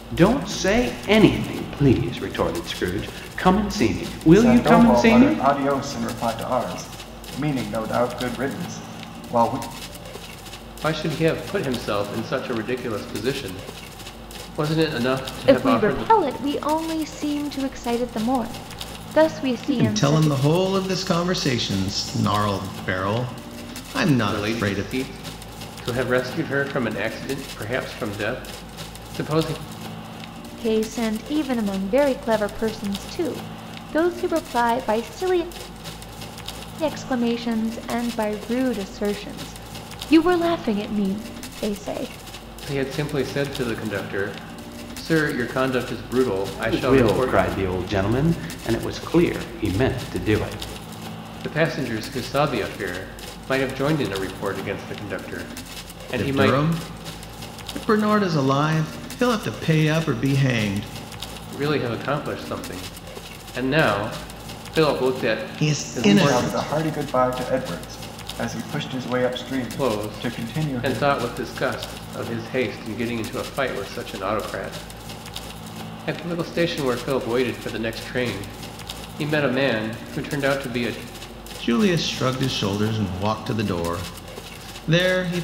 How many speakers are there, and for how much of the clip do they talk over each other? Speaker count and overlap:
5, about 9%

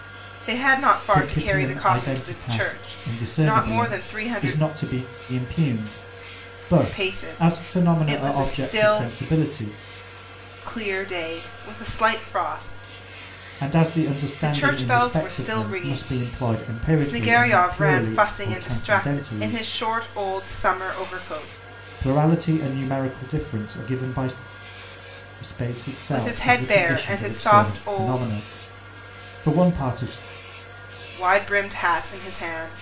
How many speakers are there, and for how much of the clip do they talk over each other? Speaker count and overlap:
2, about 37%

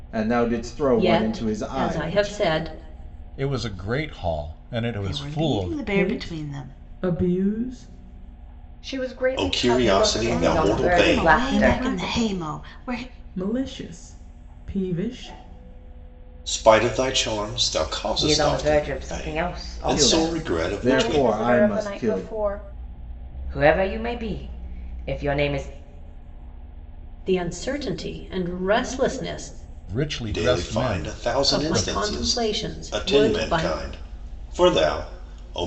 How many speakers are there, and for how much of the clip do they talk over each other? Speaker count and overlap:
8, about 37%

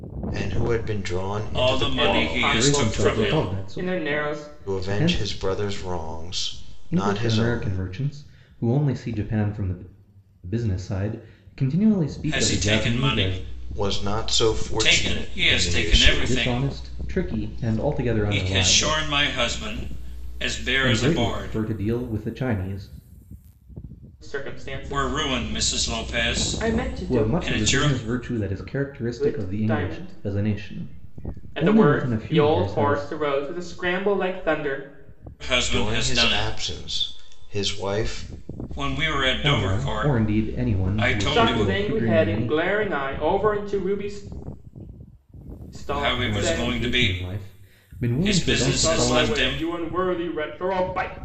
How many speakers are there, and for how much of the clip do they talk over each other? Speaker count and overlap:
4, about 50%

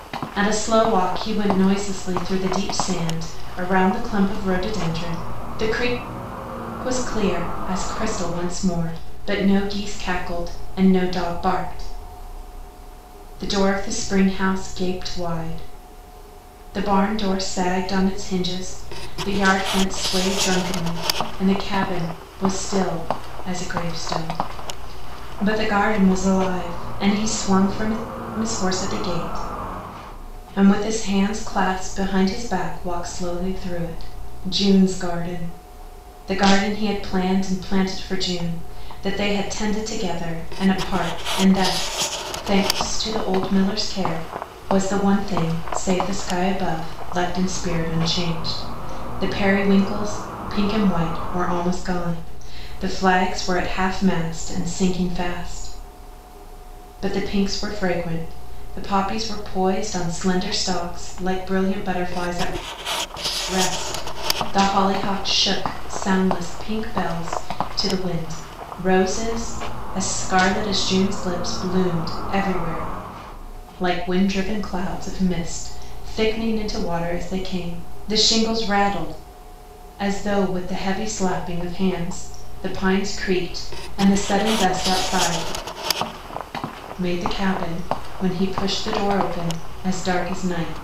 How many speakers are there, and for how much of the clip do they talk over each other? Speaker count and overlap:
1, no overlap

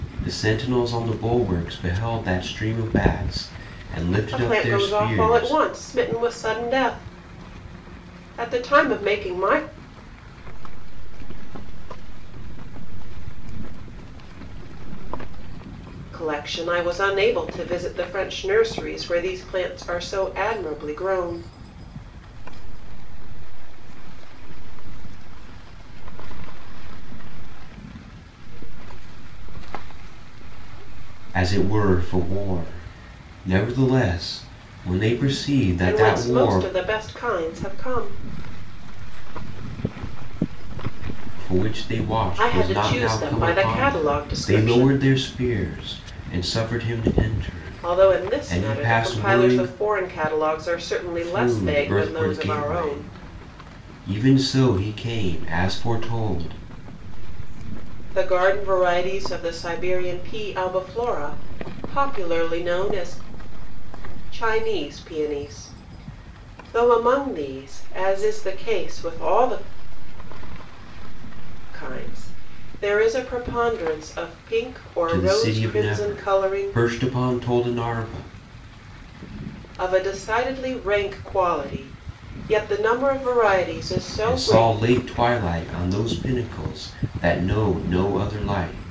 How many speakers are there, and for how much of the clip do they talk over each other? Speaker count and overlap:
3, about 27%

